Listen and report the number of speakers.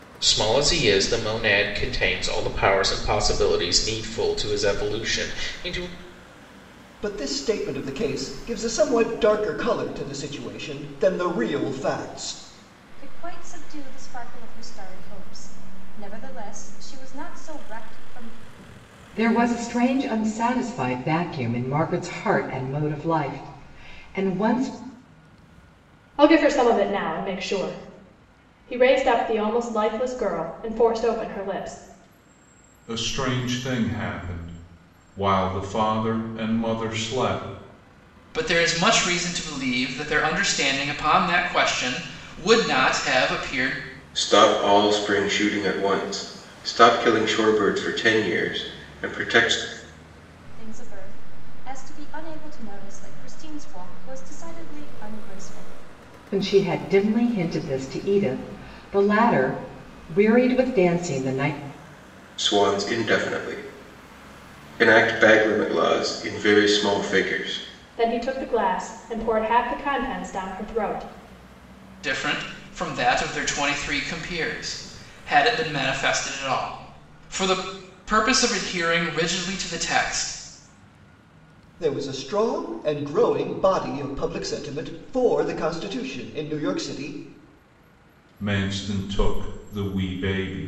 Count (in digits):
8